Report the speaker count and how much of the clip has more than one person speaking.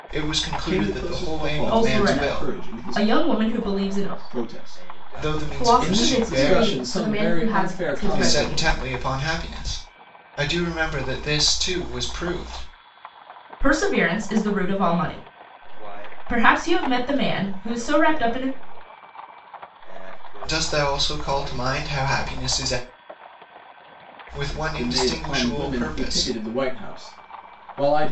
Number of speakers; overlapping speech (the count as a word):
four, about 47%